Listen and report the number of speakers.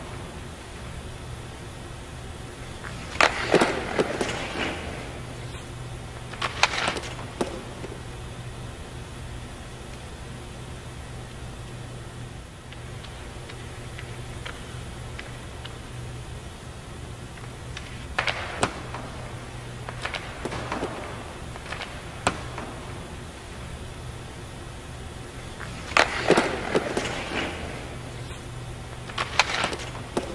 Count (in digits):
0